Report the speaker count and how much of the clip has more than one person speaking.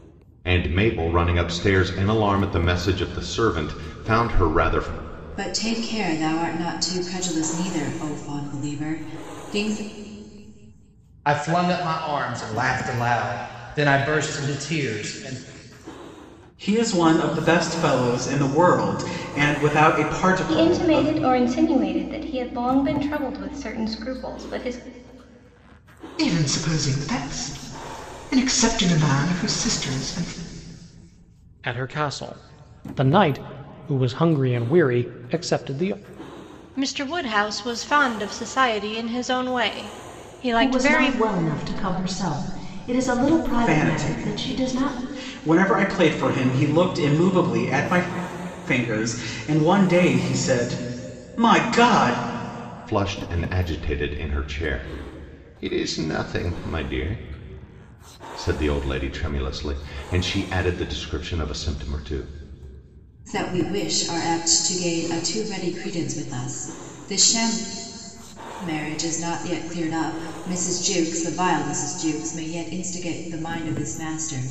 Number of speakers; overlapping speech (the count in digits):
9, about 4%